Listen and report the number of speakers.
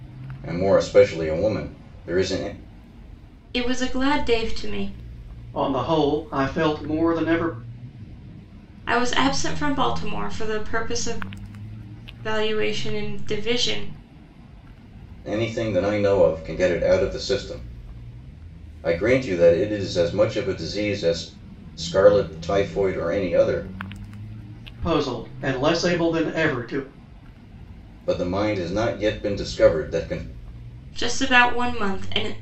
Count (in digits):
3